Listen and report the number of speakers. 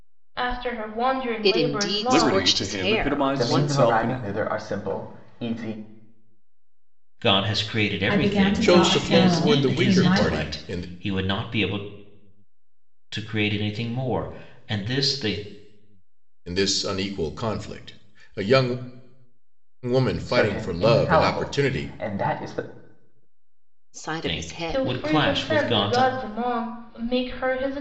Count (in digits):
7